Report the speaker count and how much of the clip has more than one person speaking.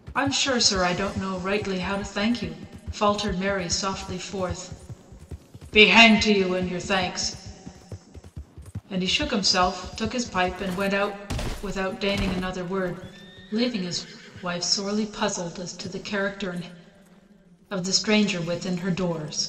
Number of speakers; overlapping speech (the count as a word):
one, no overlap